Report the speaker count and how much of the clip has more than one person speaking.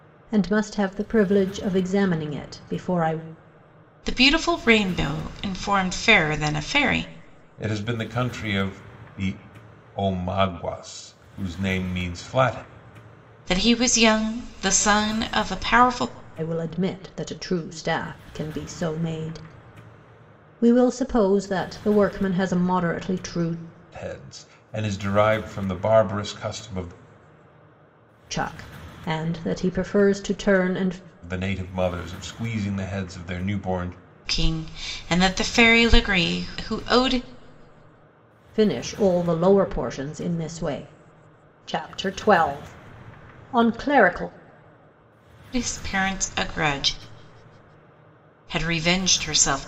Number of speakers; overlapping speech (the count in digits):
3, no overlap